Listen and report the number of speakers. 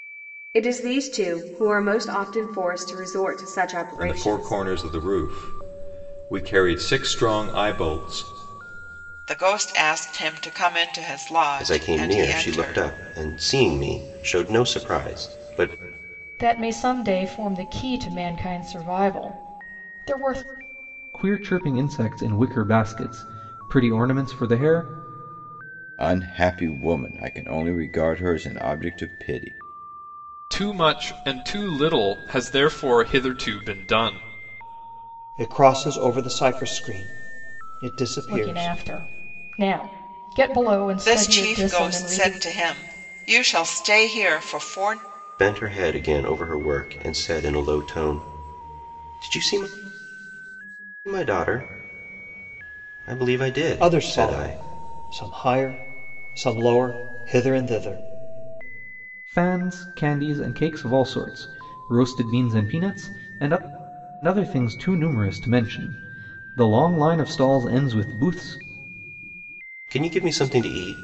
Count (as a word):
nine